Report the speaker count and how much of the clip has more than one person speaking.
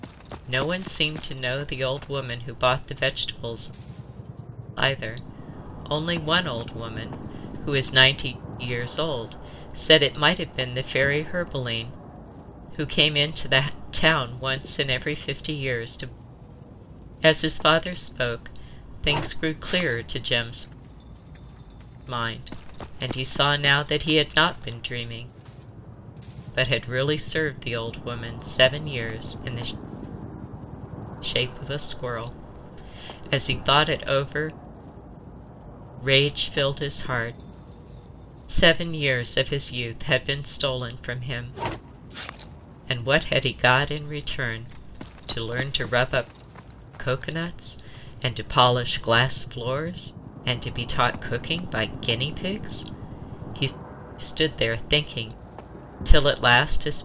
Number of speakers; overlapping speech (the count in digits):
1, no overlap